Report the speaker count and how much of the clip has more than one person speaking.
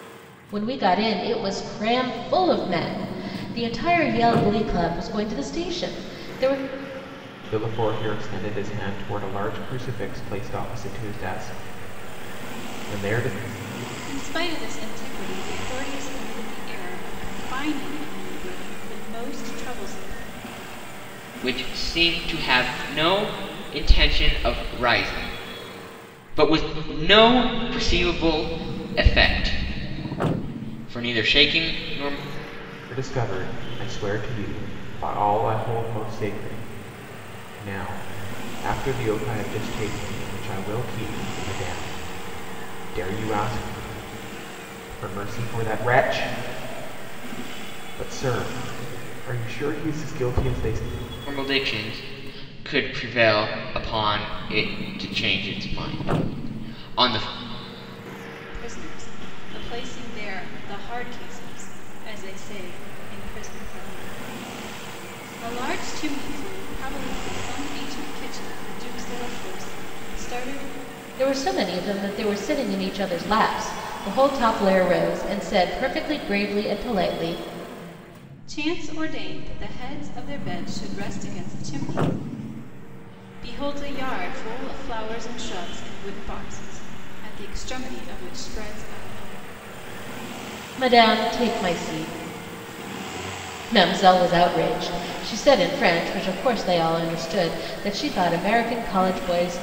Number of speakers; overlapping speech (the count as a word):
four, no overlap